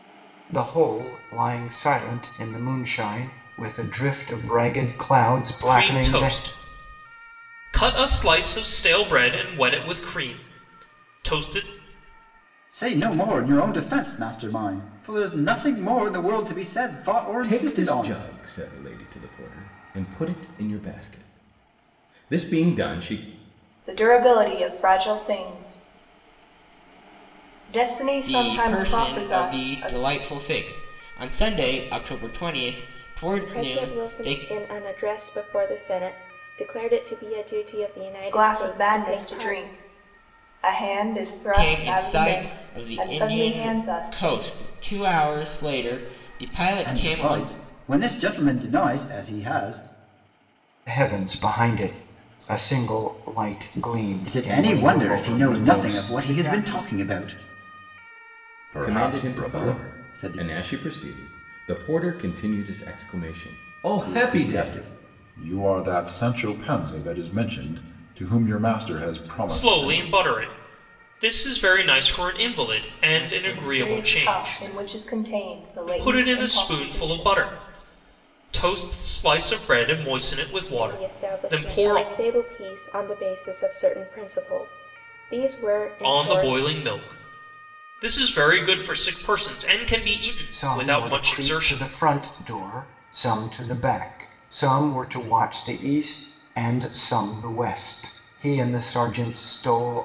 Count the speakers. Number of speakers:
seven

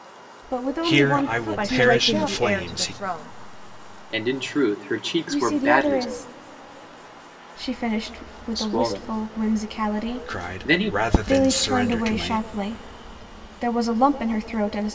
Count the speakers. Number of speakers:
four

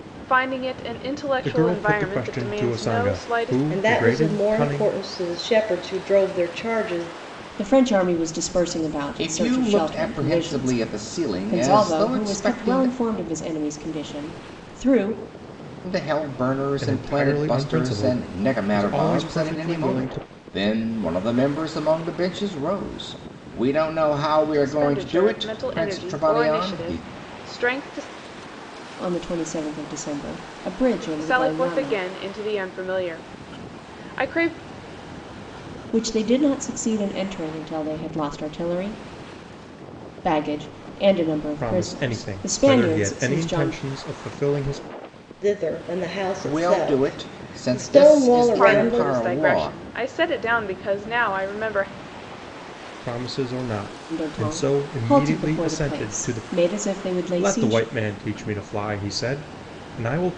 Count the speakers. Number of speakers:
five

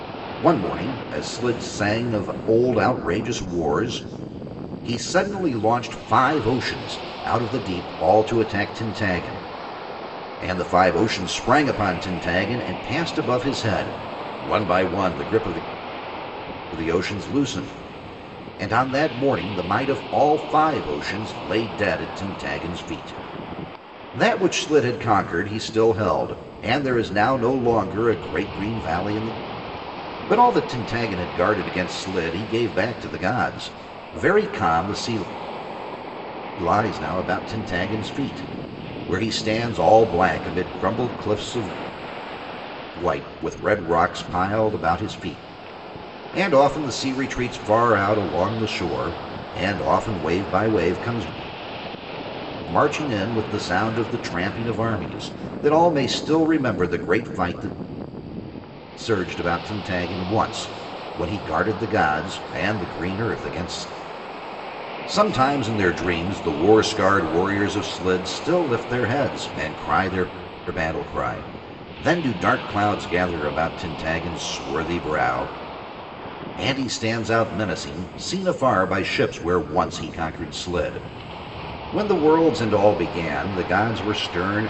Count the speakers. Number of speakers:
one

